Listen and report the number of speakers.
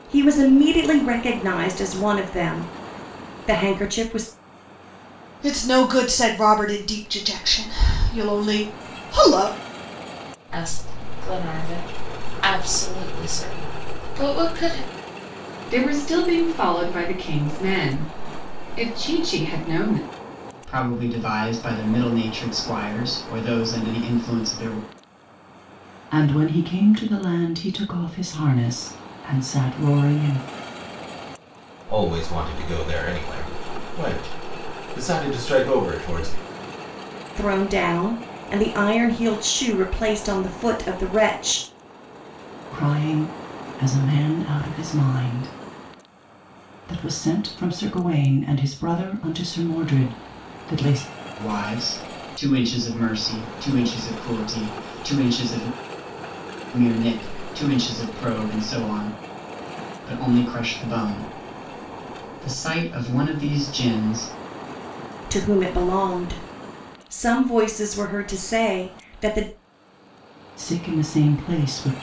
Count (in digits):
7